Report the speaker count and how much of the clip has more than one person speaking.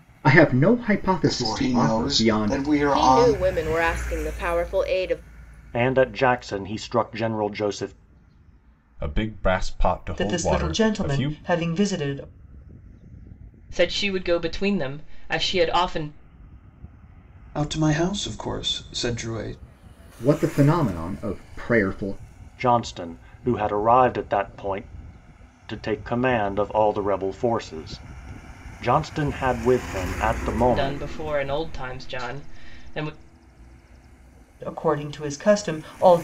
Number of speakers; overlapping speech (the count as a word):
eight, about 10%